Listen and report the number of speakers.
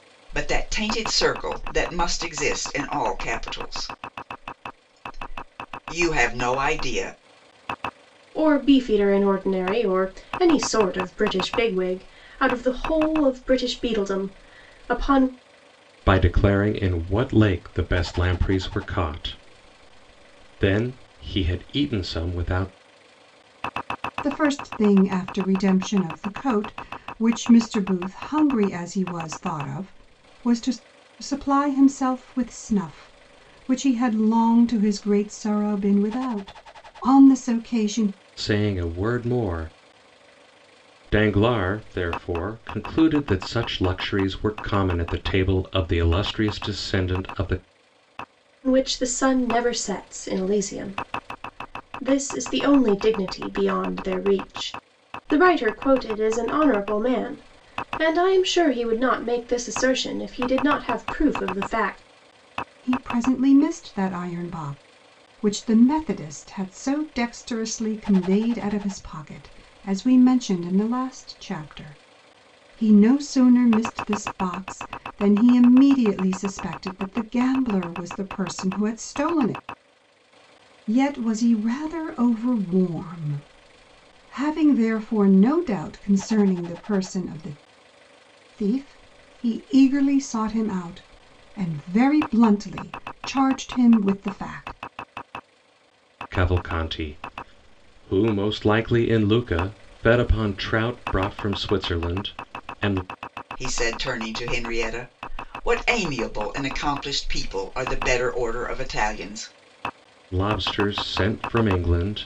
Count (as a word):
four